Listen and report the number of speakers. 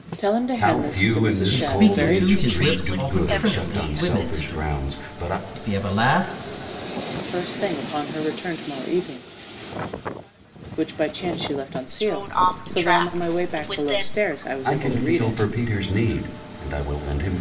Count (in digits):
4